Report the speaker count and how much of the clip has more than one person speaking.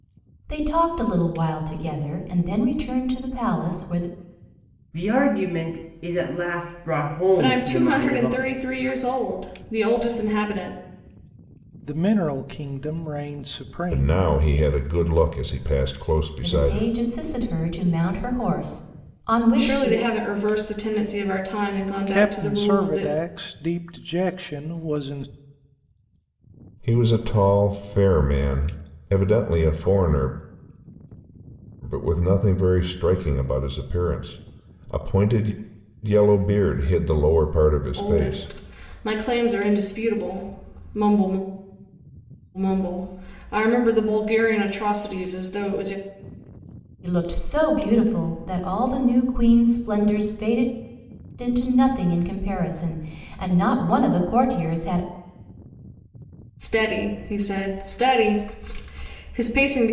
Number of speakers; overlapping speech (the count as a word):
five, about 7%